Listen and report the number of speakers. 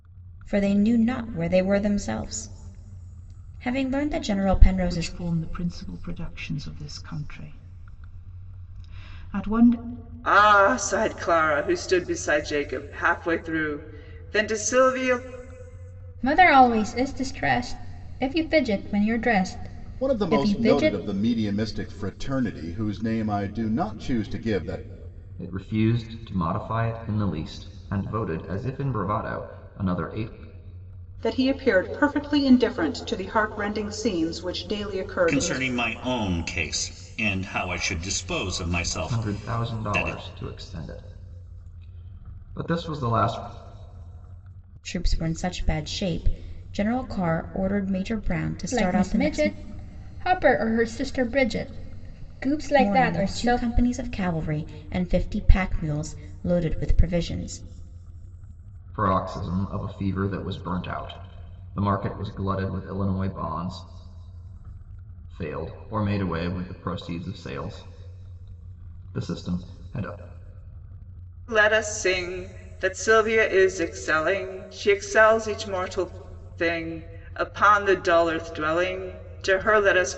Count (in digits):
8